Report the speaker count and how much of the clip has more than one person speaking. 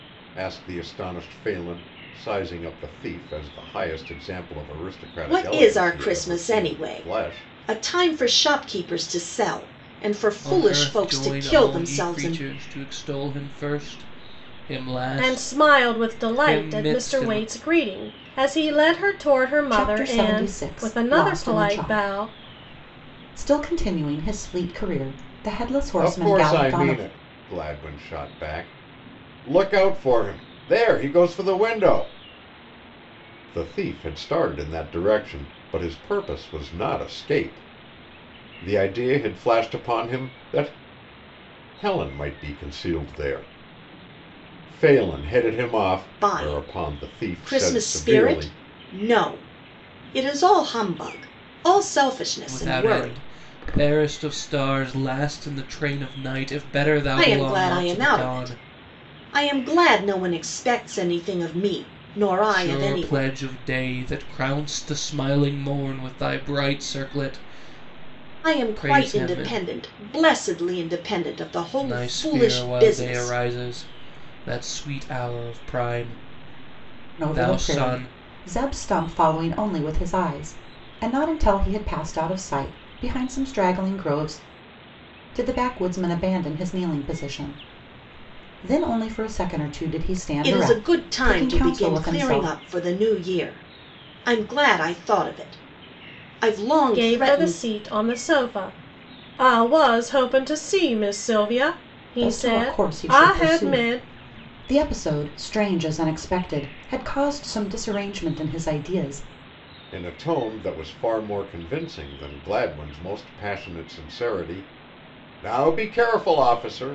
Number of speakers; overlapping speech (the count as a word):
five, about 21%